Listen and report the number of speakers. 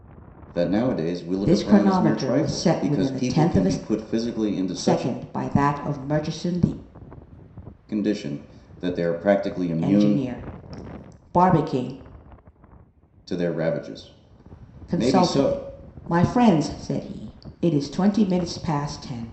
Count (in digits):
2